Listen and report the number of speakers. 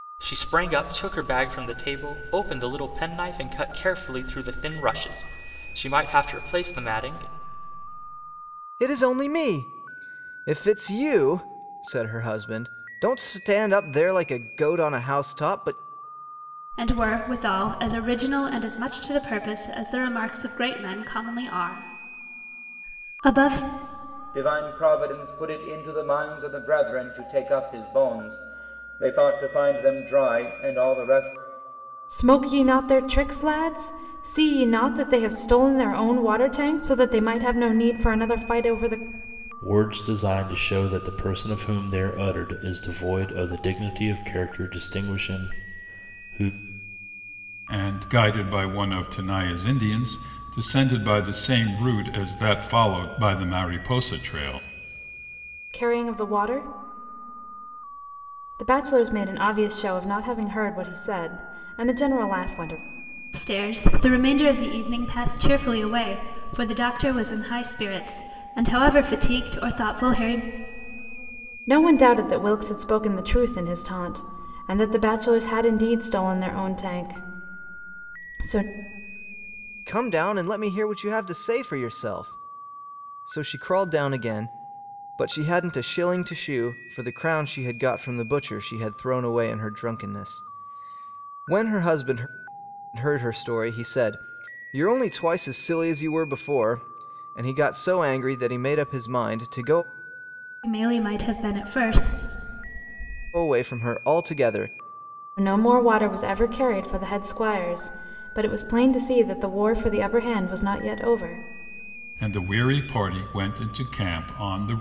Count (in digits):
7